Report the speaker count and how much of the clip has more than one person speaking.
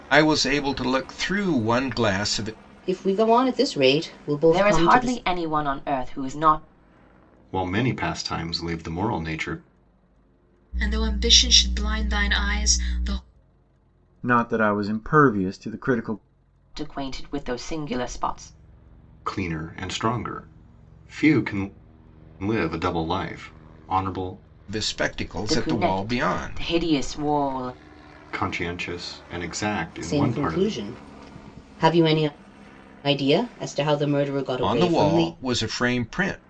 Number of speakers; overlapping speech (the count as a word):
six, about 9%